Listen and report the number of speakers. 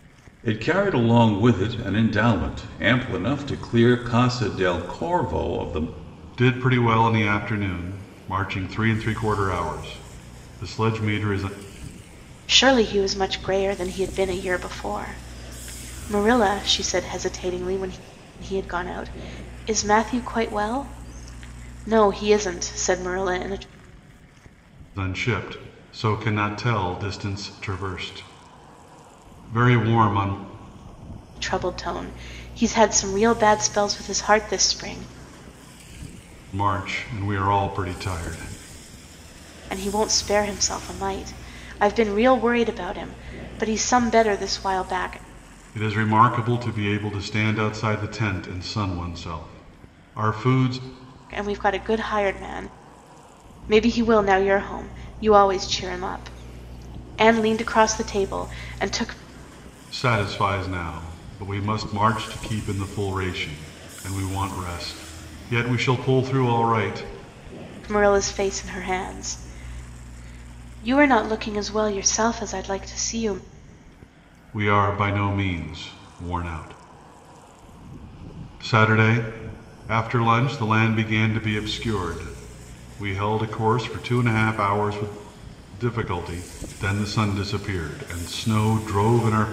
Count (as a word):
three